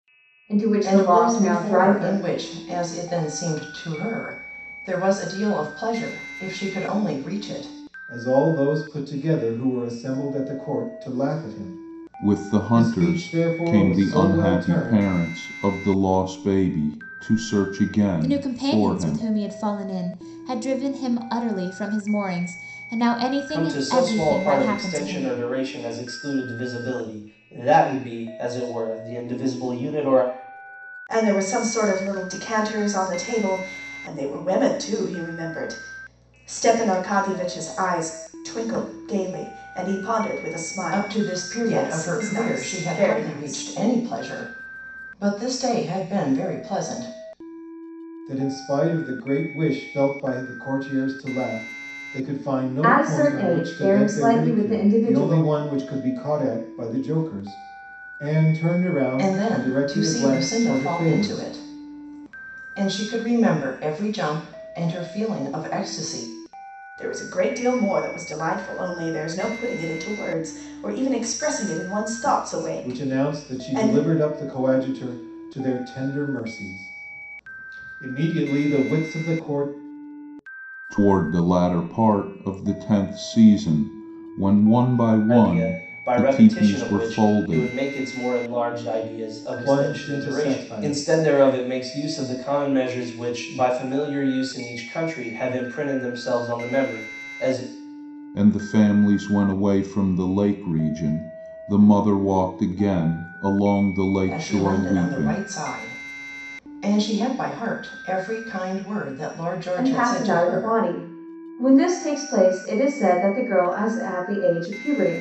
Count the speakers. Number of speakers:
7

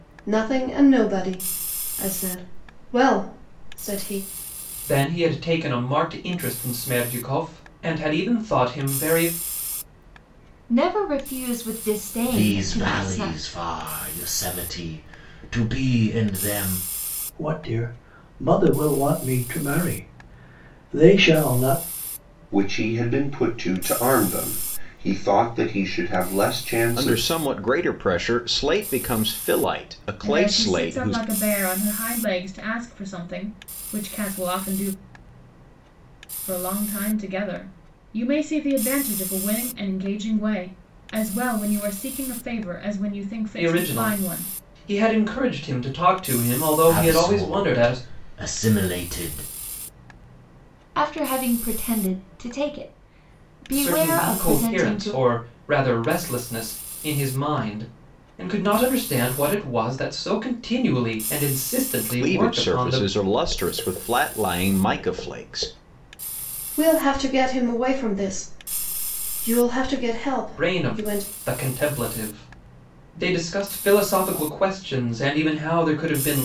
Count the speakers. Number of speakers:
8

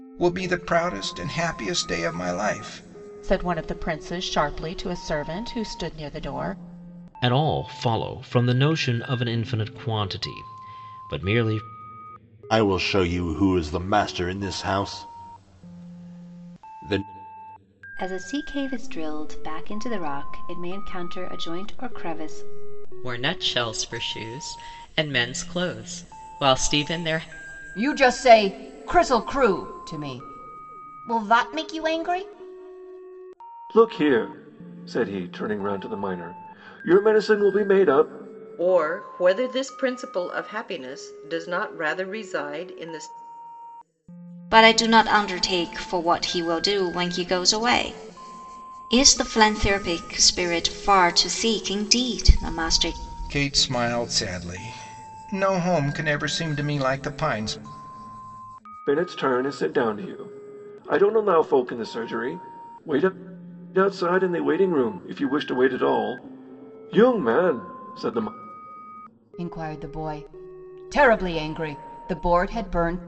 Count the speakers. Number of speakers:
10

